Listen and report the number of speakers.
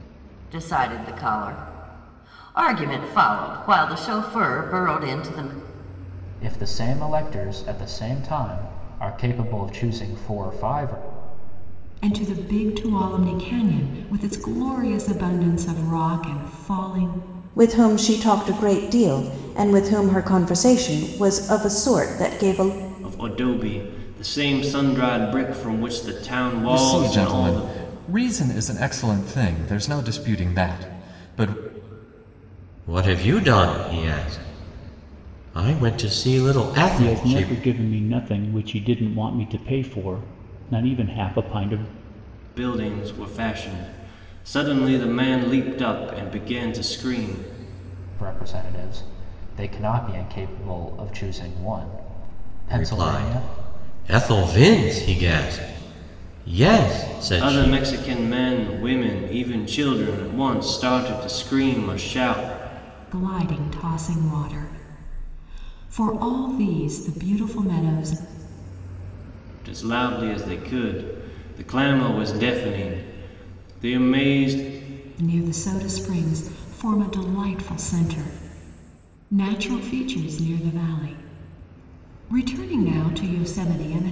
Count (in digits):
8